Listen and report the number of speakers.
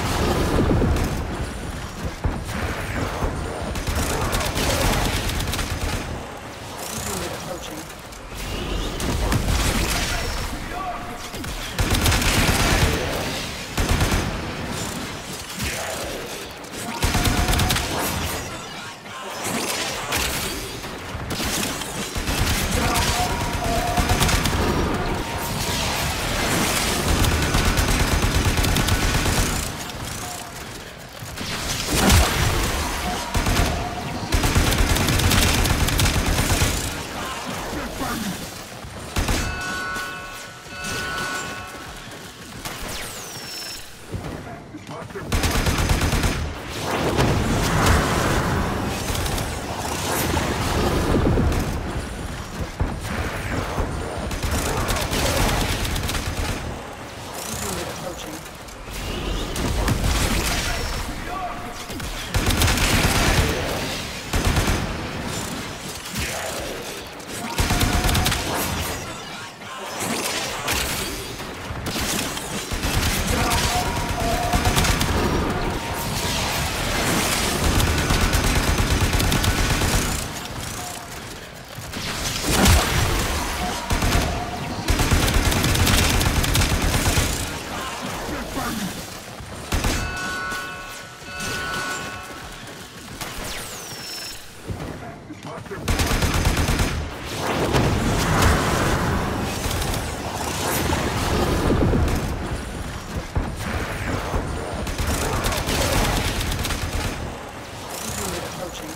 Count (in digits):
0